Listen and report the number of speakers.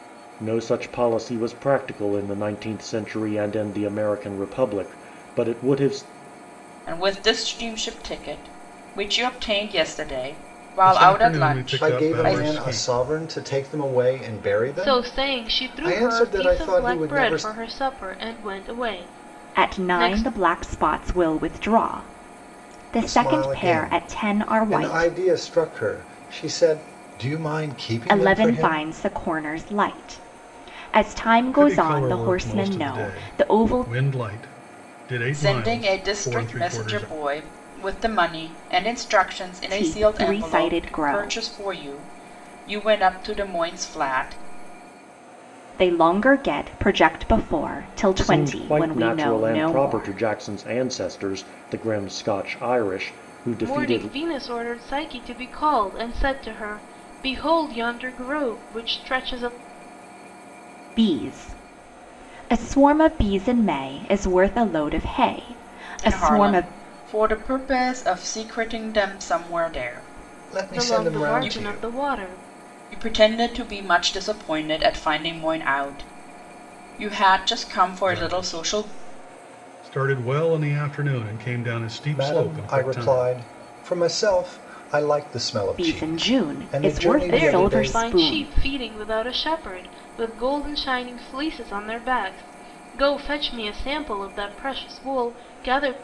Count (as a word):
six